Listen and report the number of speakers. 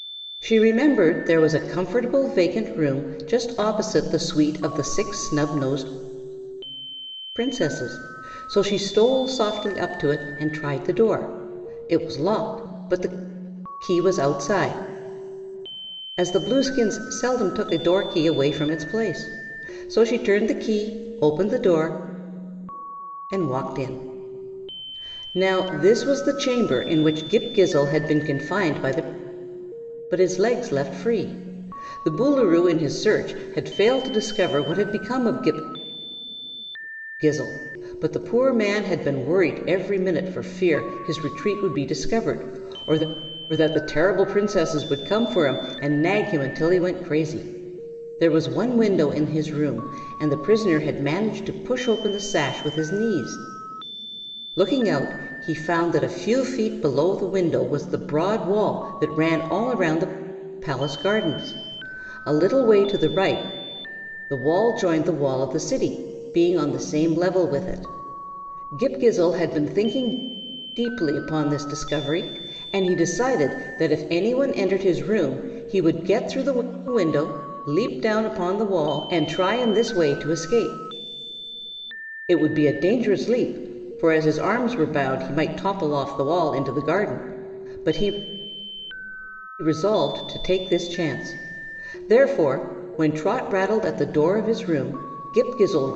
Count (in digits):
1